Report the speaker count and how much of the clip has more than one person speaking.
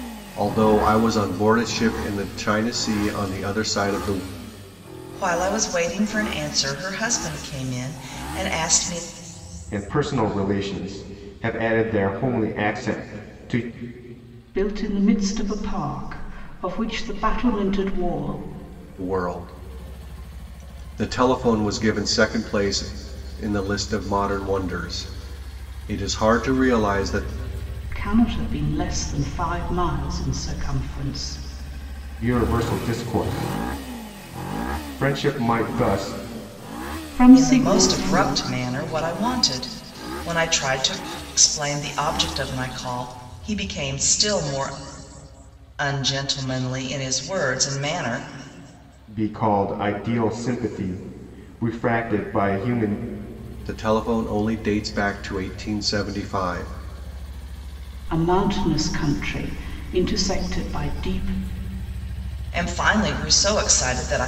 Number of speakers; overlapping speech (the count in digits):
4, about 2%